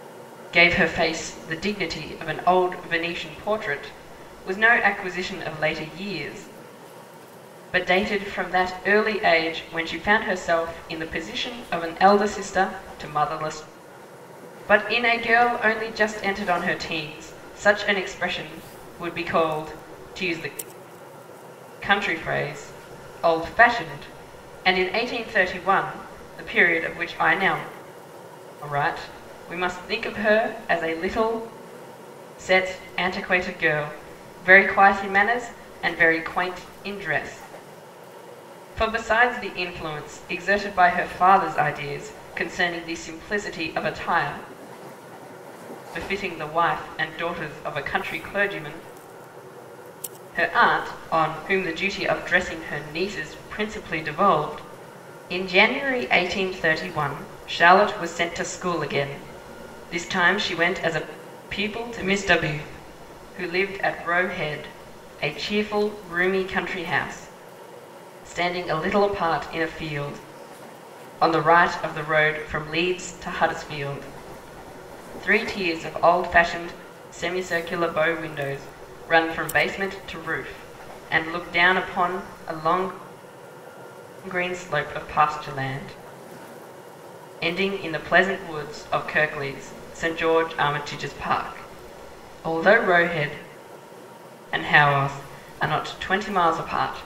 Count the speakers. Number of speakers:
1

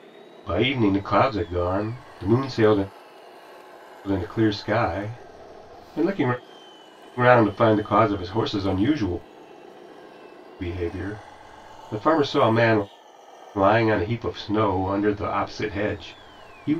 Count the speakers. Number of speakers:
1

